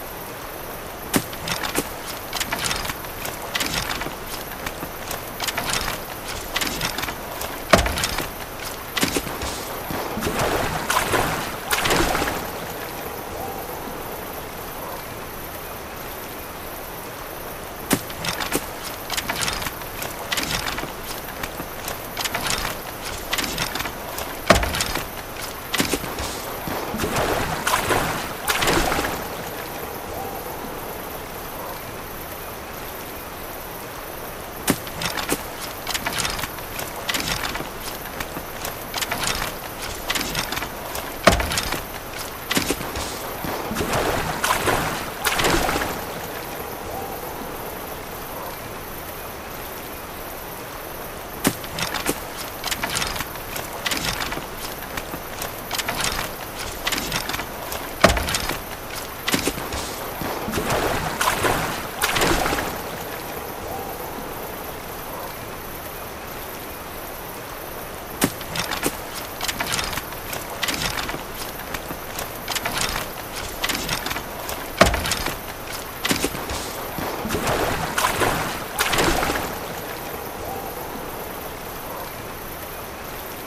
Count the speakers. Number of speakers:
0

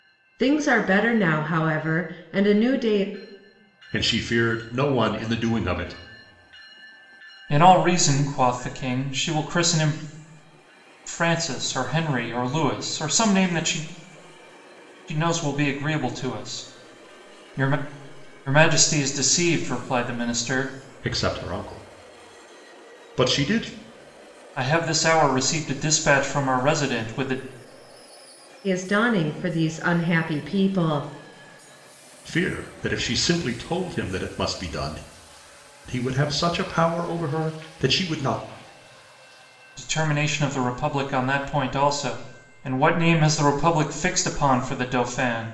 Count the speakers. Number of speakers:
3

